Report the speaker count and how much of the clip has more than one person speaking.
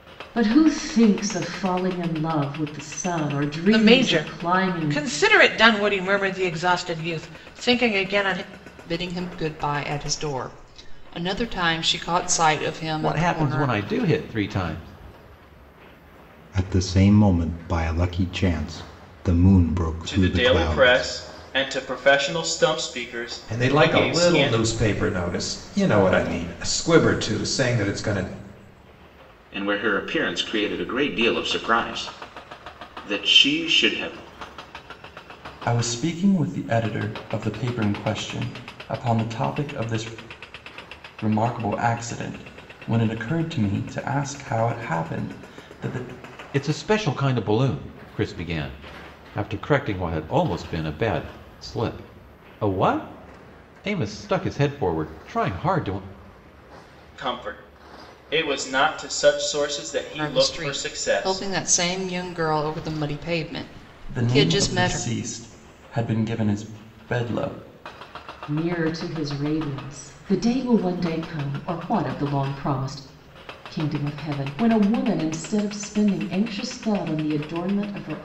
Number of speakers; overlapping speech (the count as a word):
nine, about 8%